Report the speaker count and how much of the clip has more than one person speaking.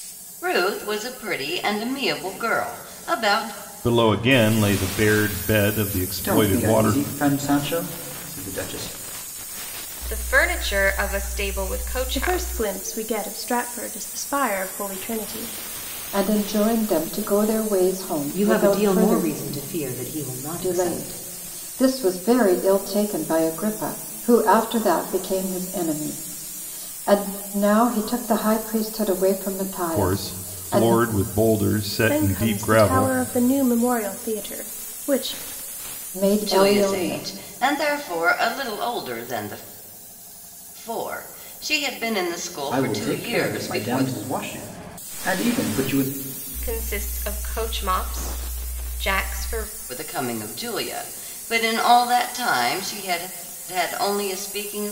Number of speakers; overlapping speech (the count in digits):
7, about 14%